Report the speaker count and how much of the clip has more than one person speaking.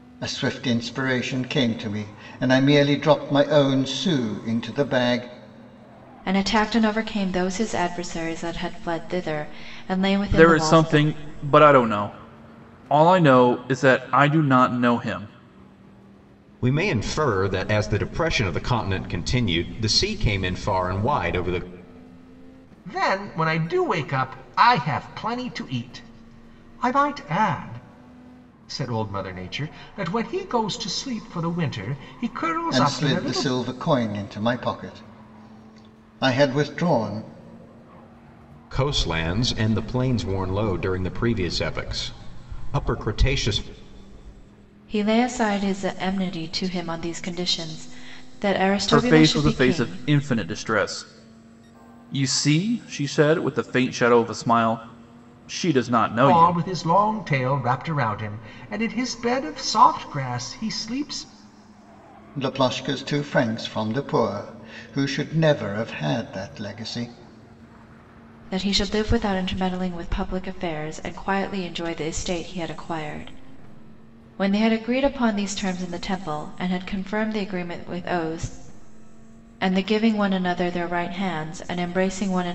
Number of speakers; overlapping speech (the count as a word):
five, about 4%